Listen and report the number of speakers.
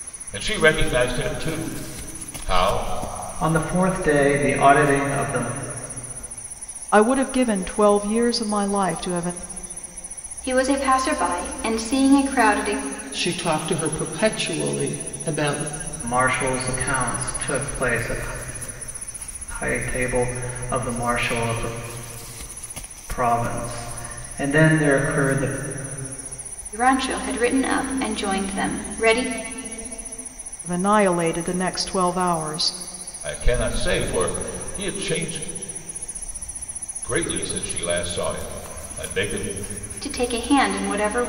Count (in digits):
5